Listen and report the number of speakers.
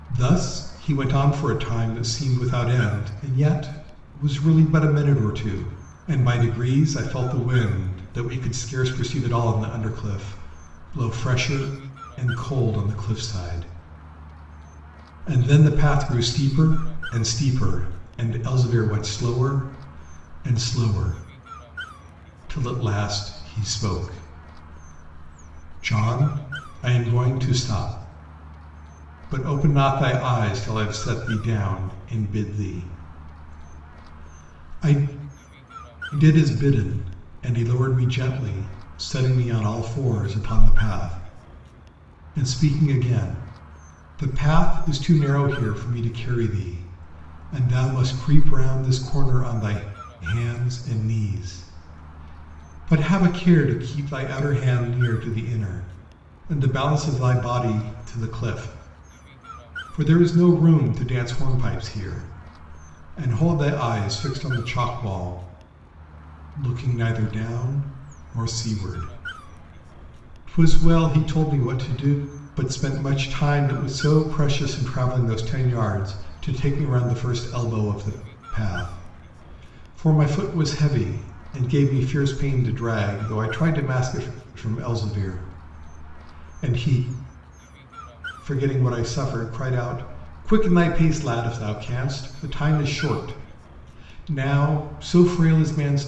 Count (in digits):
1